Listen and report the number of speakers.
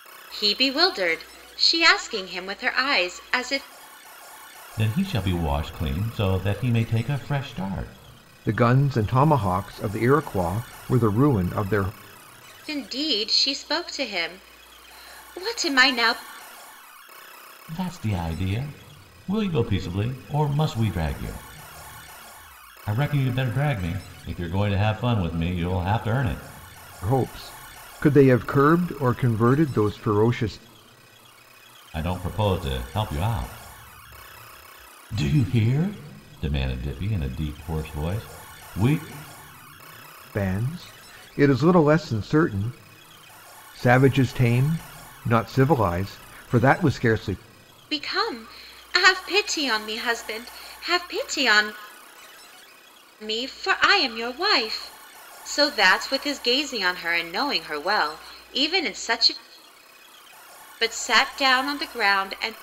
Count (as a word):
three